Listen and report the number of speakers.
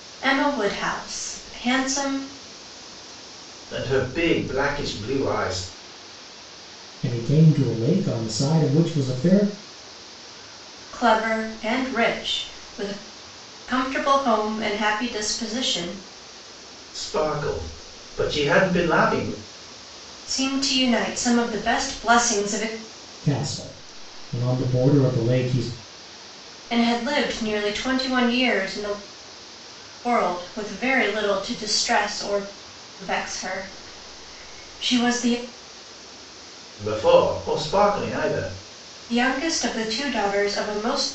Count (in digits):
3